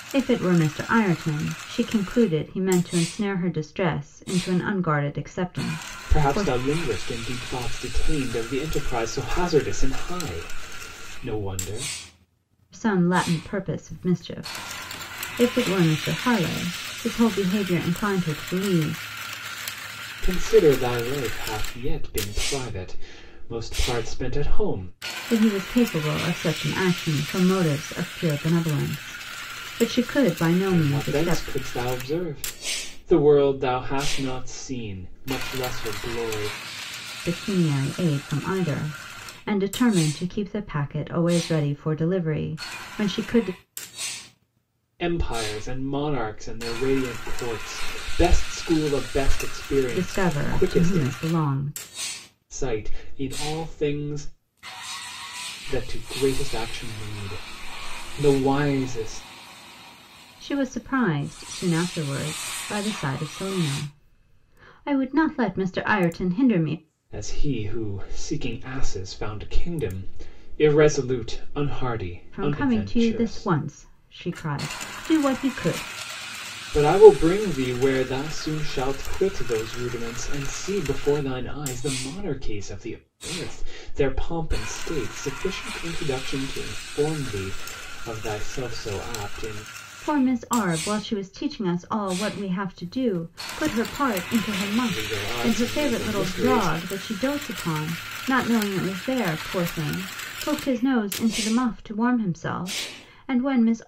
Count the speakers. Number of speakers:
two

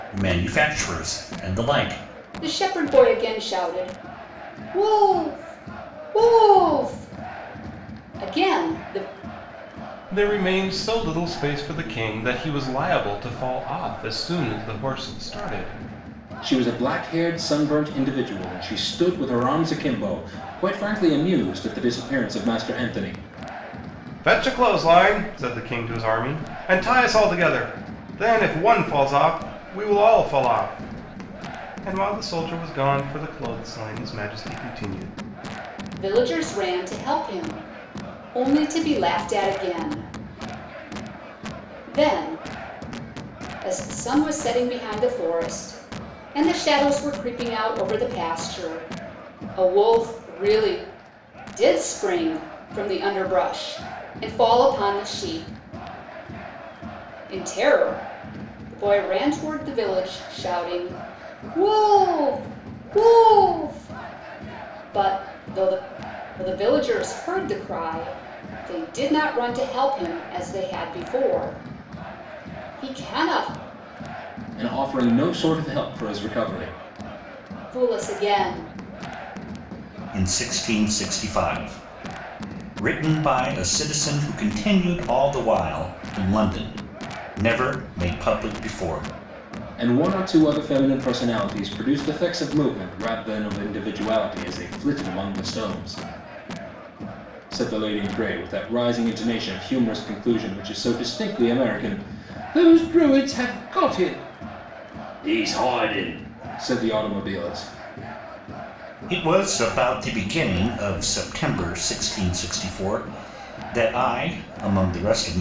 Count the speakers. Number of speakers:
four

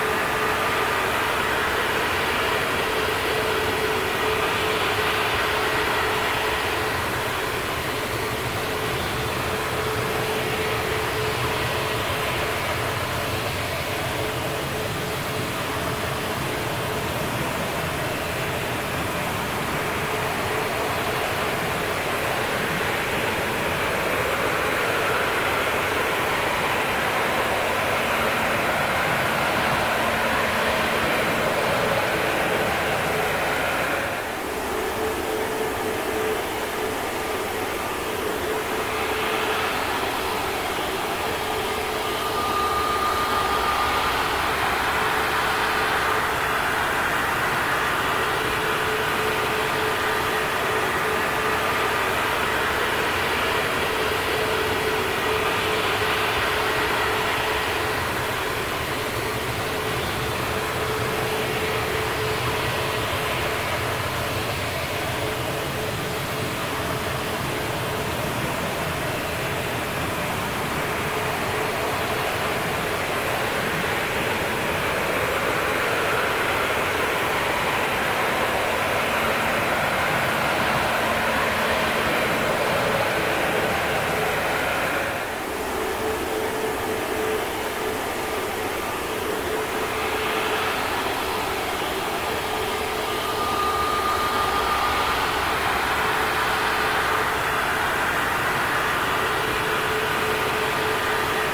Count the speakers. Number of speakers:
zero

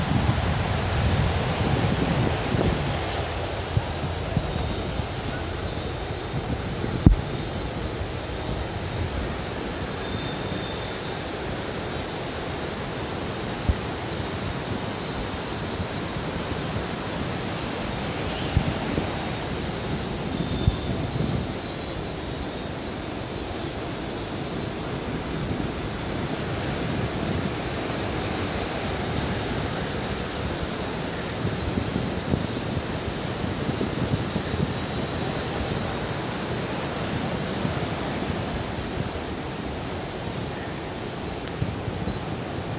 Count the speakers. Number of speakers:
zero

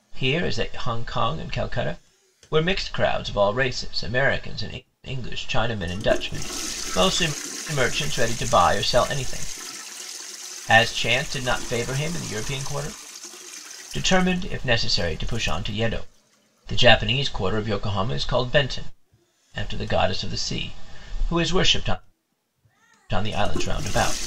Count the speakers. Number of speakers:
one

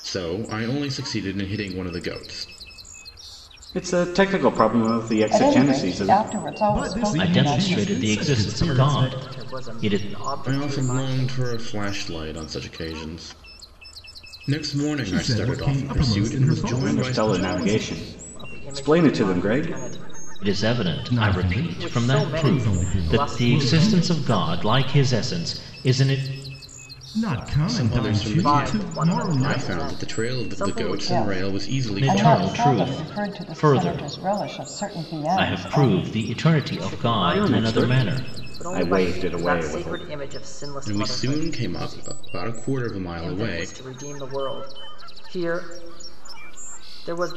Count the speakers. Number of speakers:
six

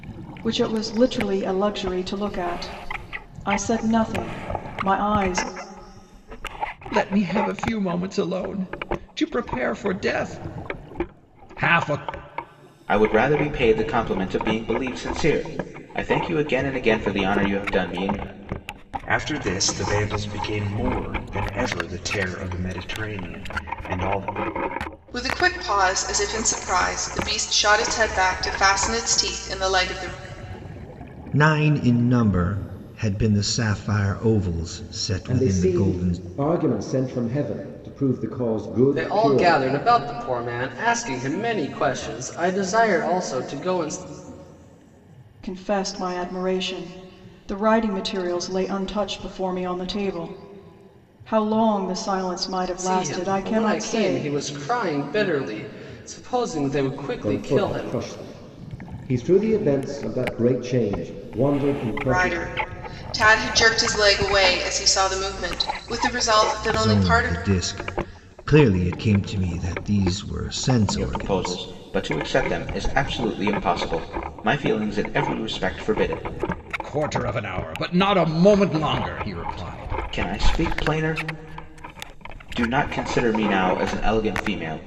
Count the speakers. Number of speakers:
eight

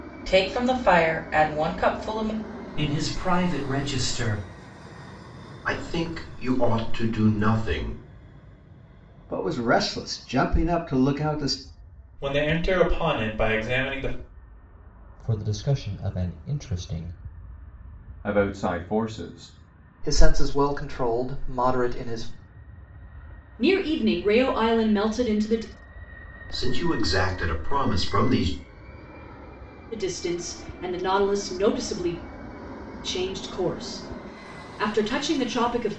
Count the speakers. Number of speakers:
nine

